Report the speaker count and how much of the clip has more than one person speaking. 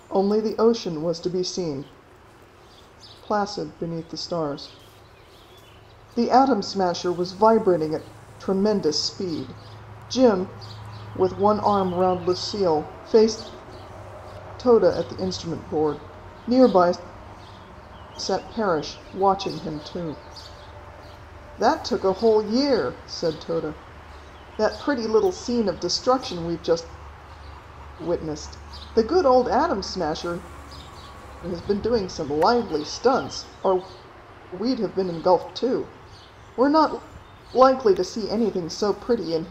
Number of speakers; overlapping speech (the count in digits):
1, no overlap